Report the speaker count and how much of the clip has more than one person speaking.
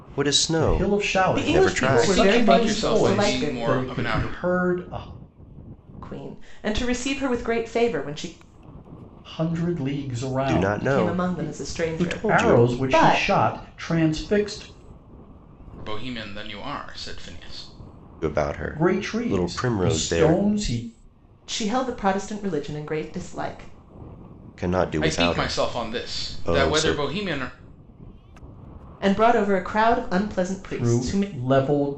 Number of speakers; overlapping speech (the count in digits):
4, about 35%